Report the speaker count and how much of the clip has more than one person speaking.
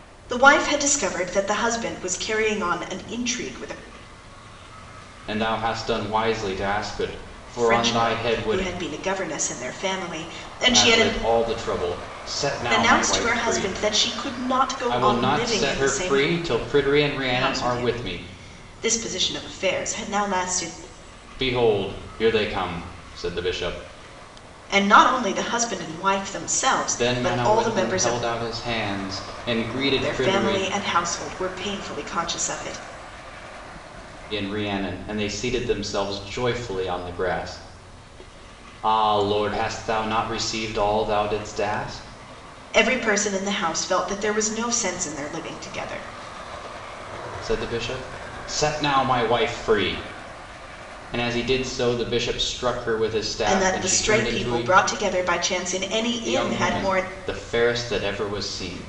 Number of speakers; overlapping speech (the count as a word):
two, about 15%